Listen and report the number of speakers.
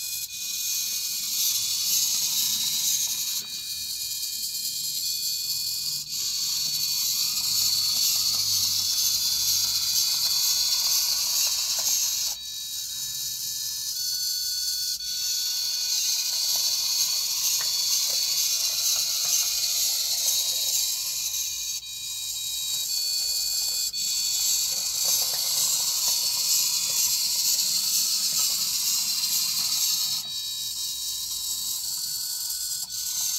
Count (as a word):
zero